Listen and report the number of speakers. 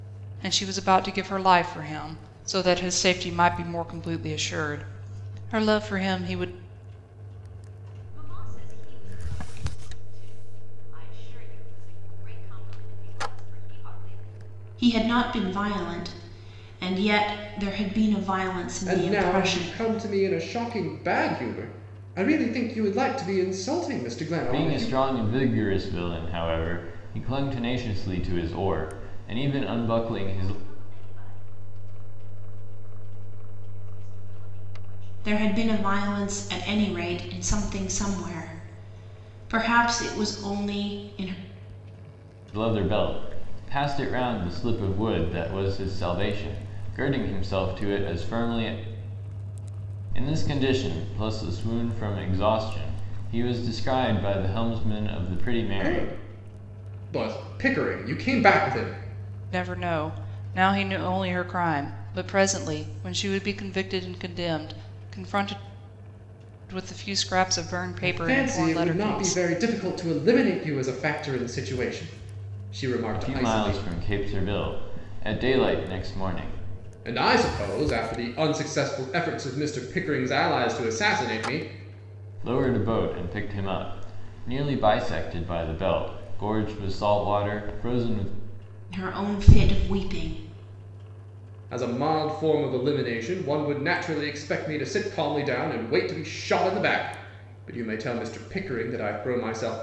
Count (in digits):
5